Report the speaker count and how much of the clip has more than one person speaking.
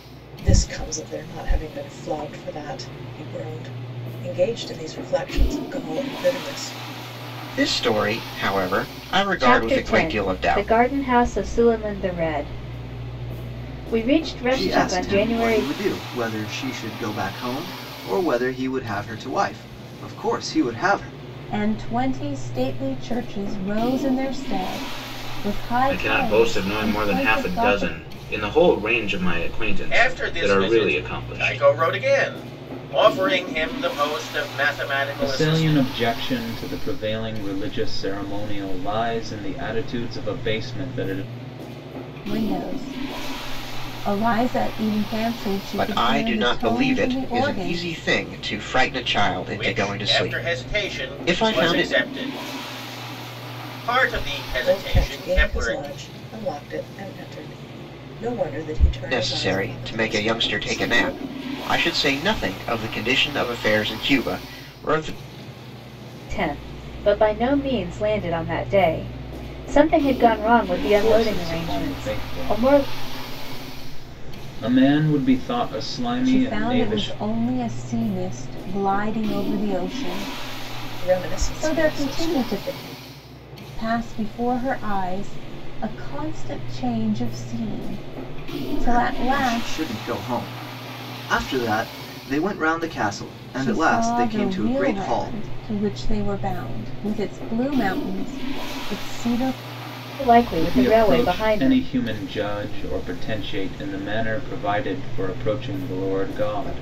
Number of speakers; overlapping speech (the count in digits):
8, about 23%